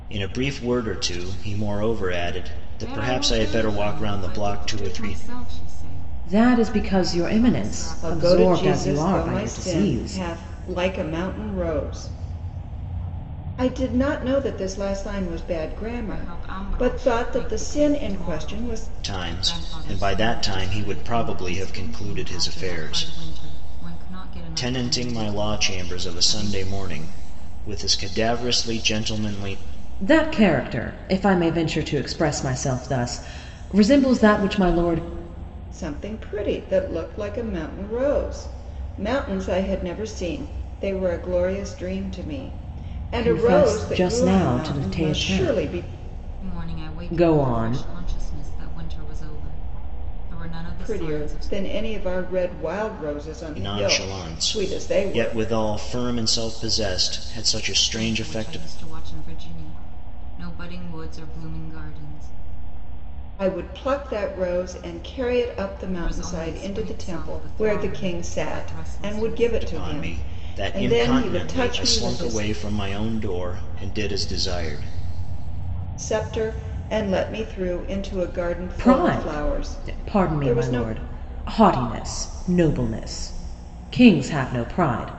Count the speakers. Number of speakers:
four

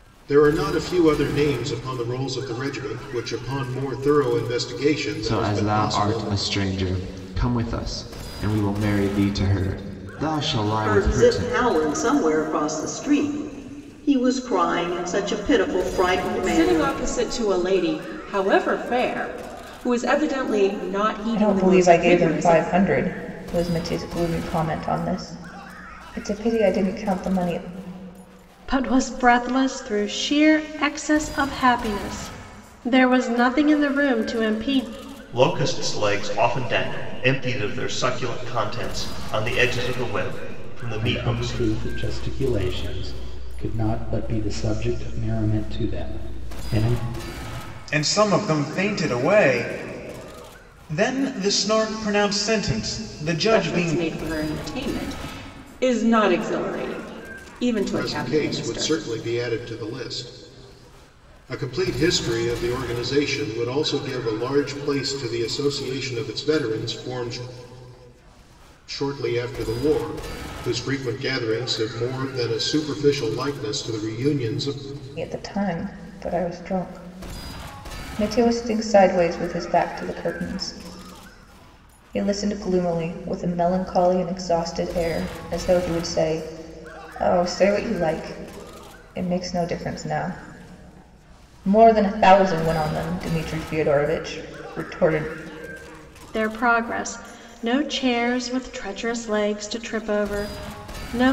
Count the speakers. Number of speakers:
nine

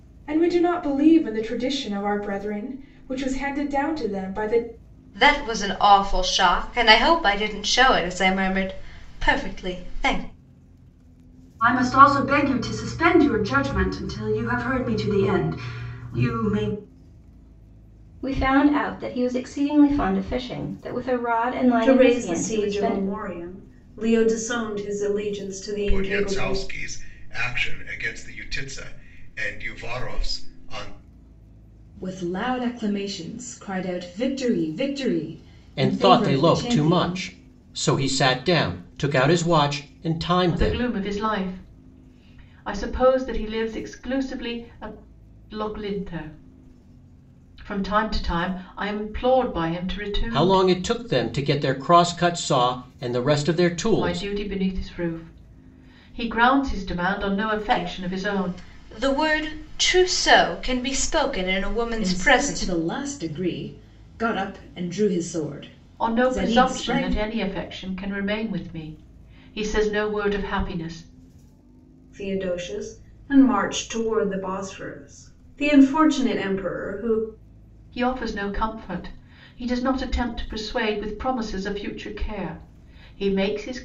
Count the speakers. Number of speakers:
nine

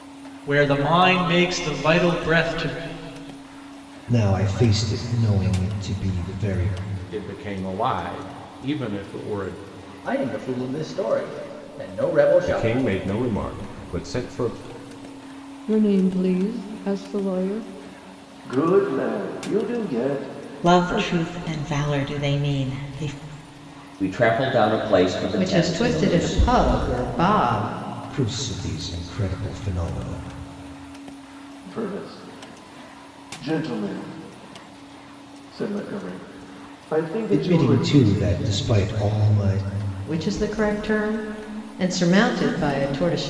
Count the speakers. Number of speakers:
ten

